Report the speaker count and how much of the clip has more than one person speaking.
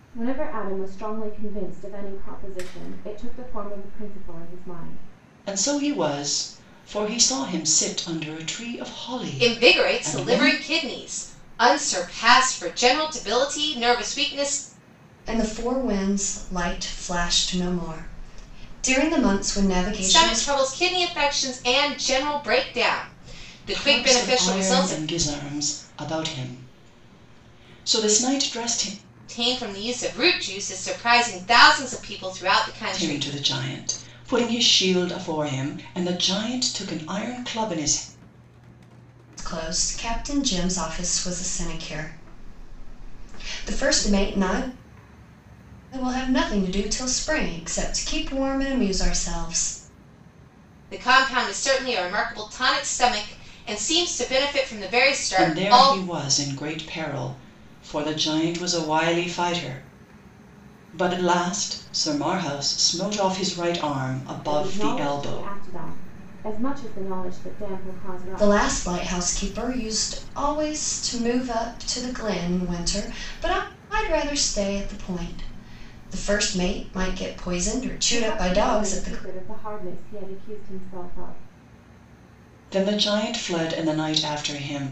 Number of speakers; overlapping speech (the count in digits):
4, about 8%